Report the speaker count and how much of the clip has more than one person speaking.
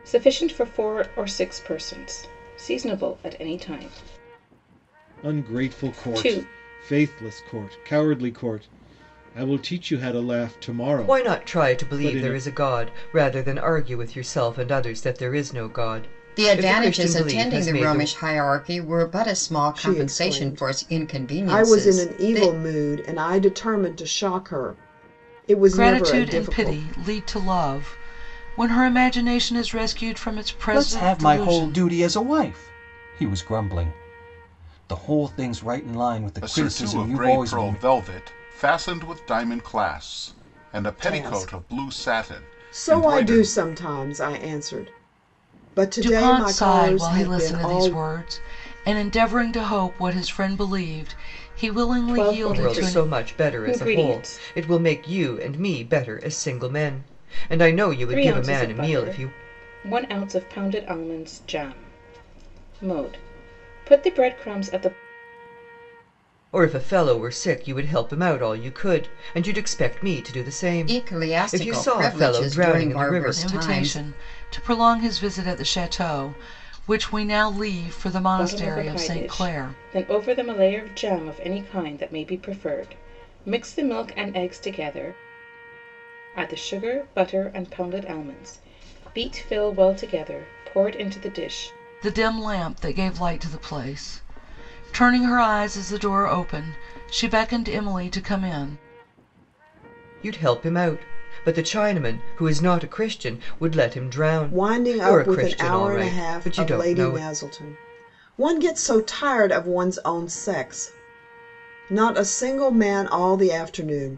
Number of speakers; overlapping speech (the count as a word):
eight, about 23%